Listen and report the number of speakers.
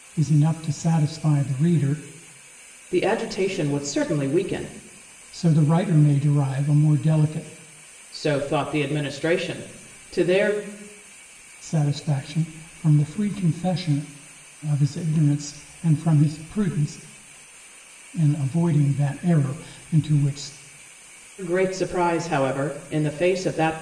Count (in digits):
2